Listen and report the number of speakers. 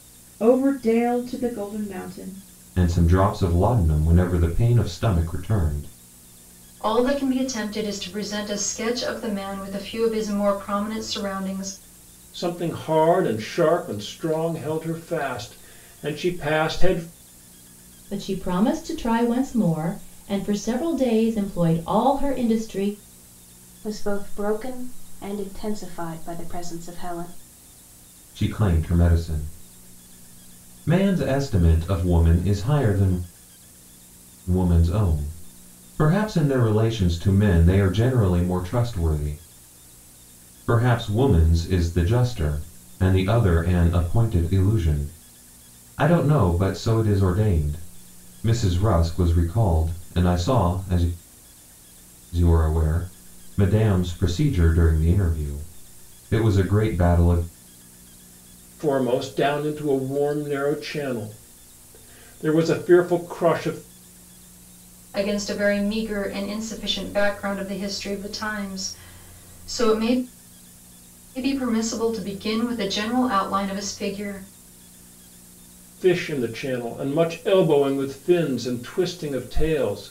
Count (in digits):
6